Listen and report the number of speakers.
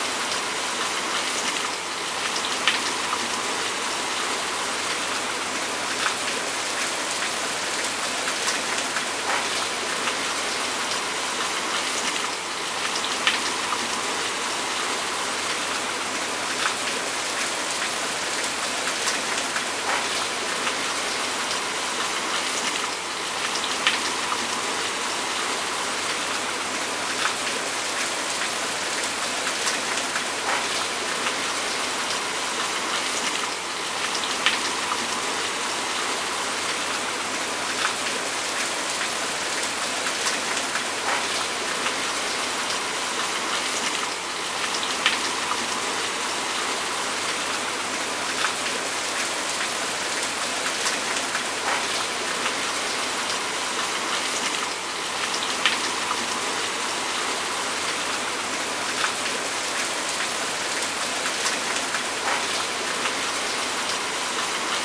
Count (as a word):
zero